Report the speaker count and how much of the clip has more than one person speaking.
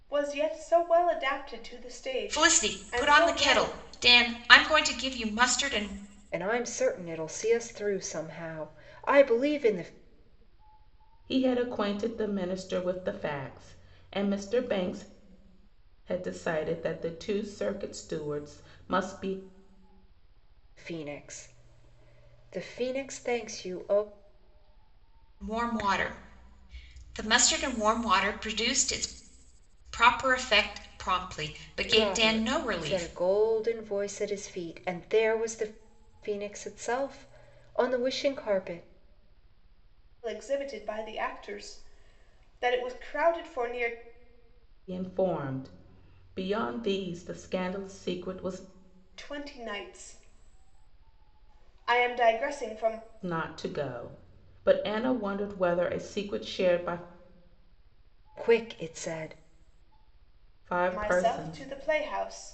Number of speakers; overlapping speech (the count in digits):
4, about 6%